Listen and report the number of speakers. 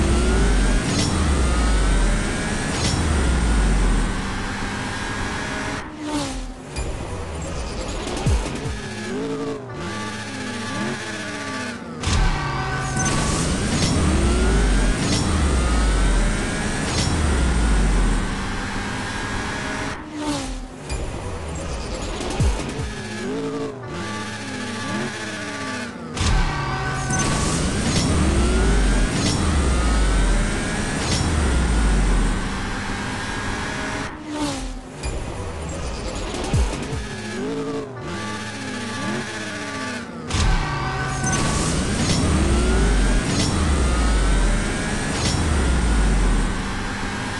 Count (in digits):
0